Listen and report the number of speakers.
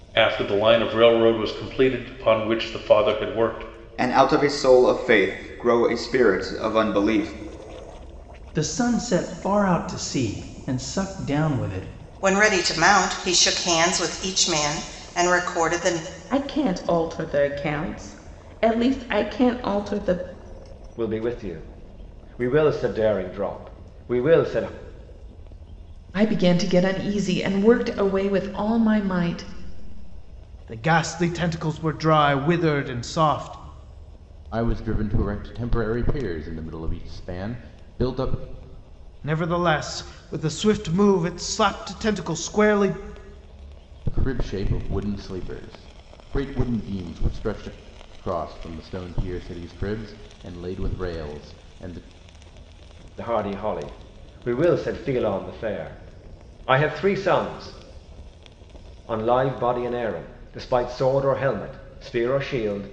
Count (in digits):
9